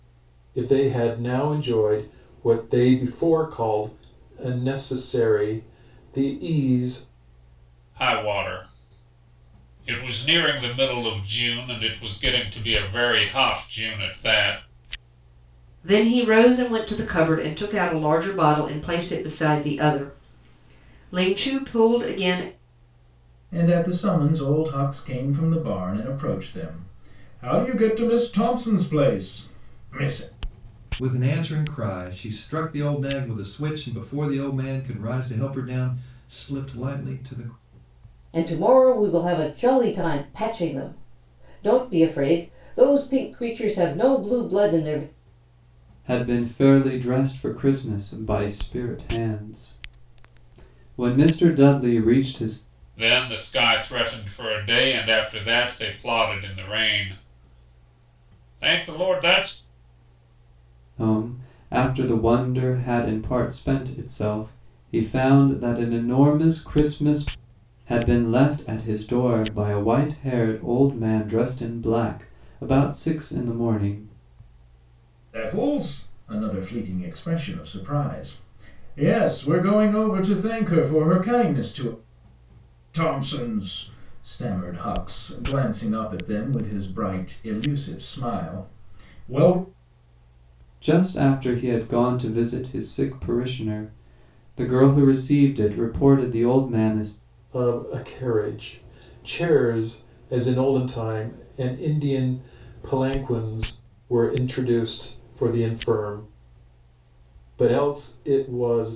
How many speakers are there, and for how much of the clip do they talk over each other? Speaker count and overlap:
7, no overlap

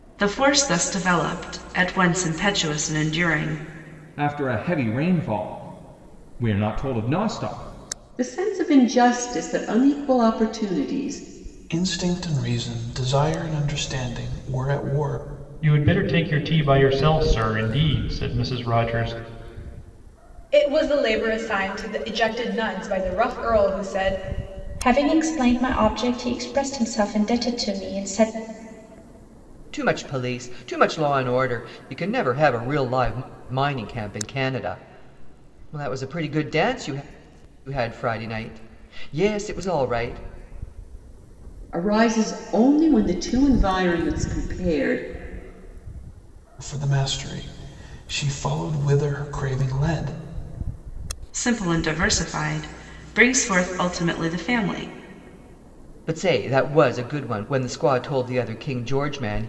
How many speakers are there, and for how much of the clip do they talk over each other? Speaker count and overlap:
8, no overlap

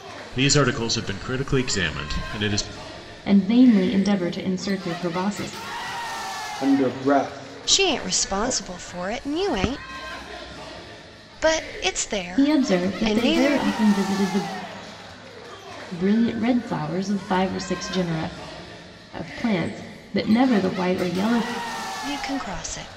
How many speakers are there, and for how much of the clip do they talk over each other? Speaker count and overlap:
4, about 11%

